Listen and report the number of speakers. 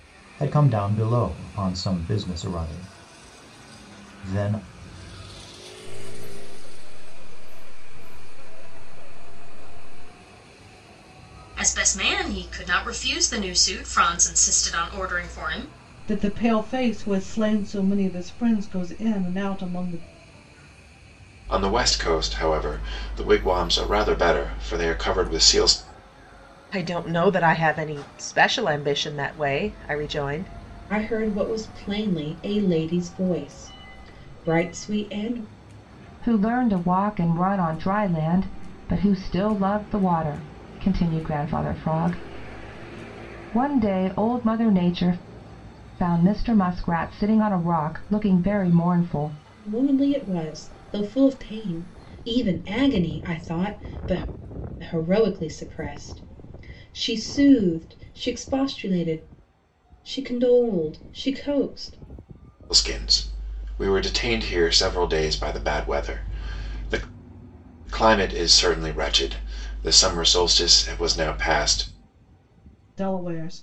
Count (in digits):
8